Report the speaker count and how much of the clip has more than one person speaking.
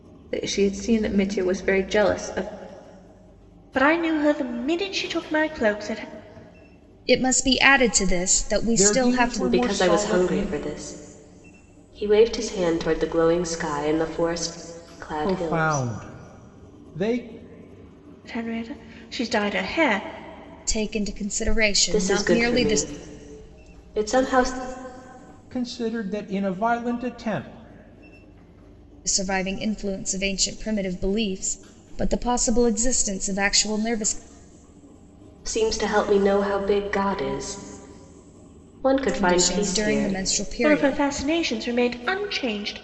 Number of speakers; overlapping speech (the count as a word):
five, about 12%